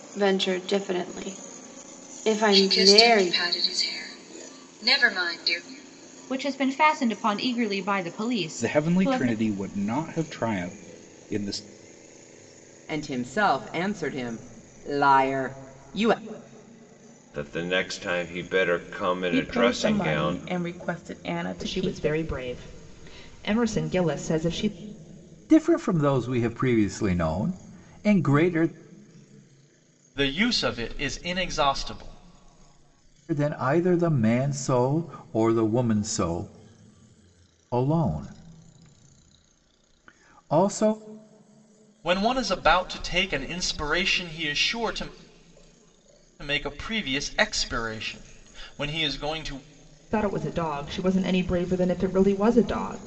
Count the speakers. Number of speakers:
ten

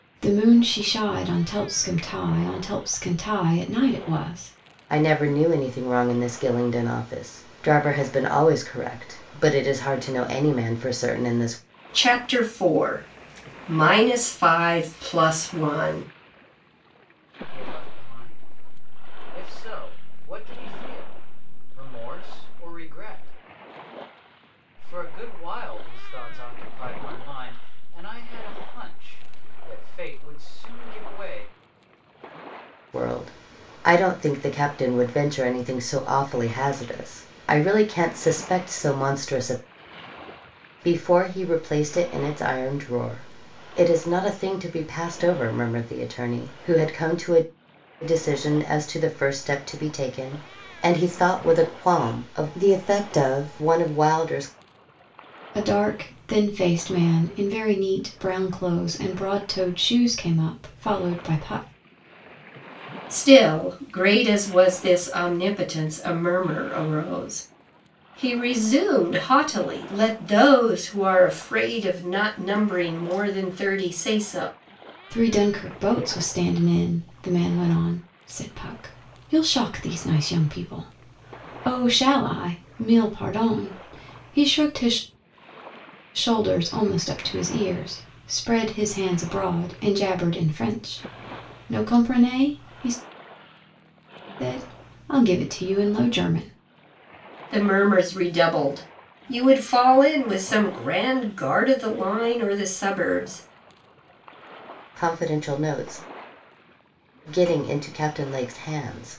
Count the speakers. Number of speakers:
four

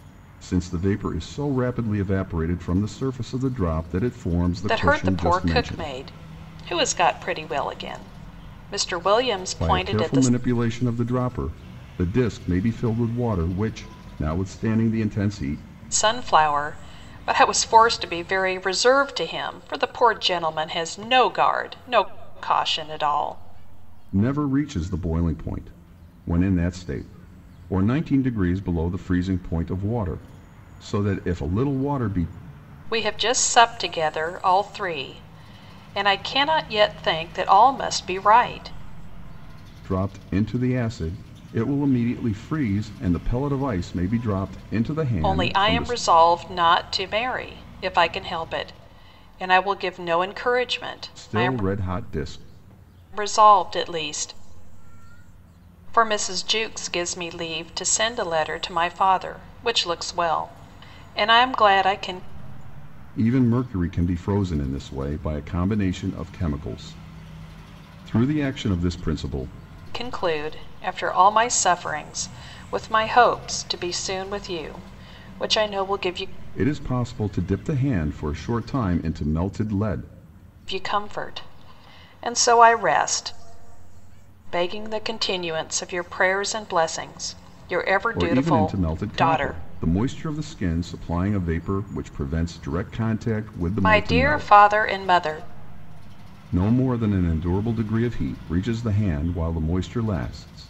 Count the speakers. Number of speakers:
two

